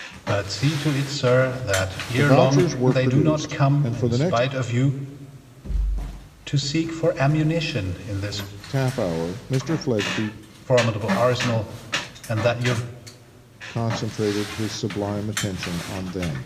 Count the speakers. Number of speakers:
2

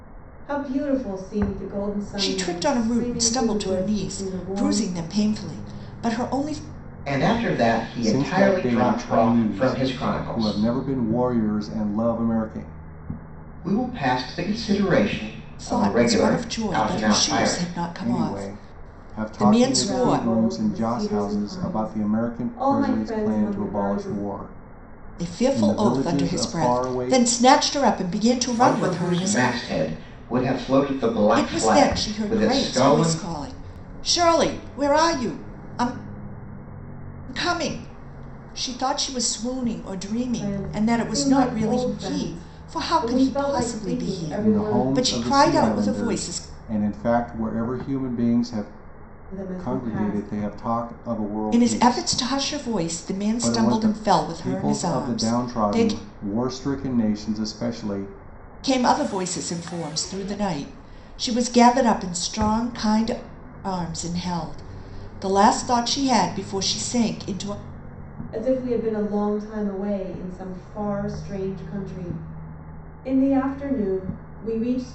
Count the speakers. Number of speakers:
4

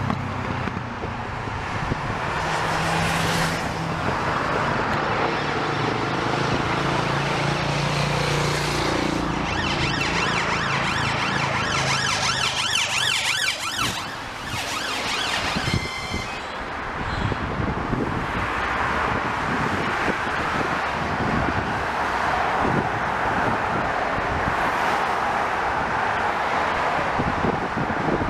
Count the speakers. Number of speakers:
0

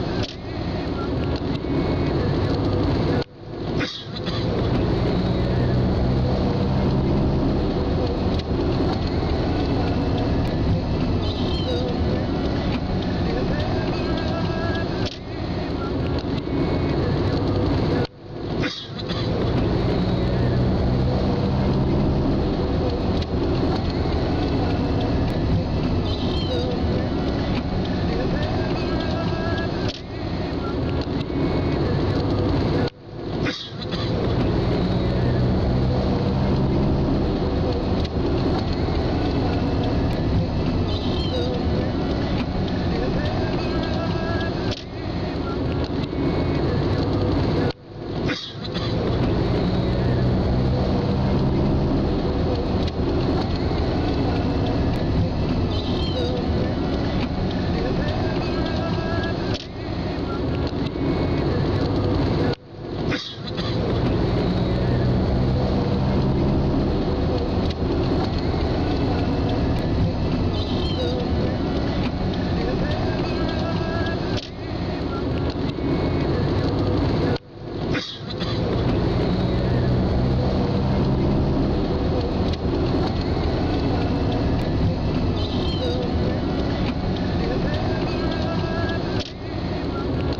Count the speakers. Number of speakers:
0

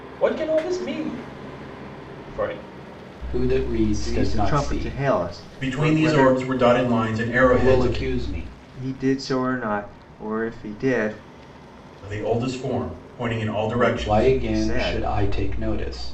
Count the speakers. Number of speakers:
4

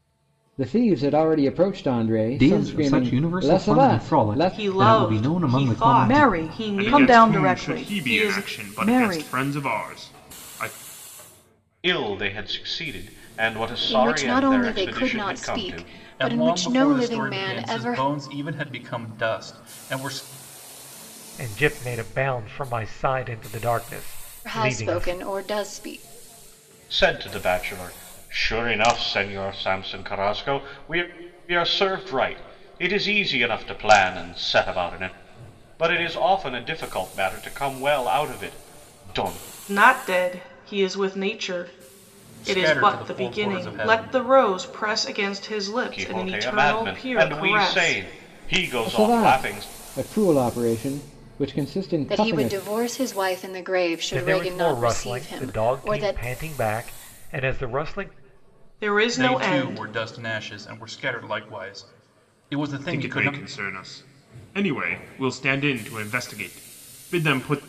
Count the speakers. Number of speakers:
9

